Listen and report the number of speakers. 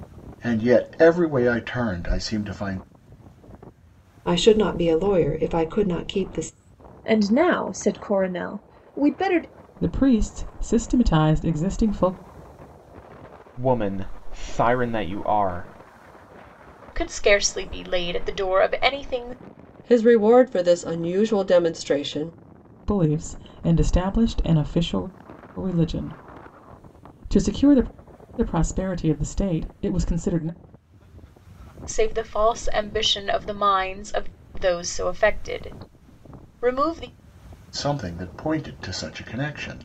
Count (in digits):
7